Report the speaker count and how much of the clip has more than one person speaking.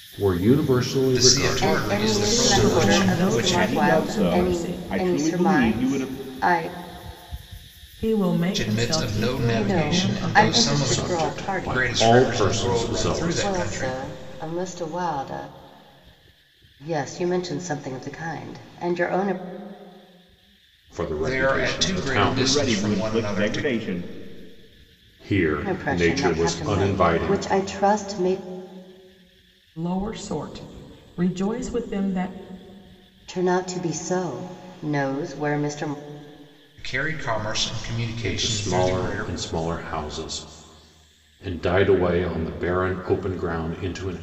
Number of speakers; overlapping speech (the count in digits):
5, about 36%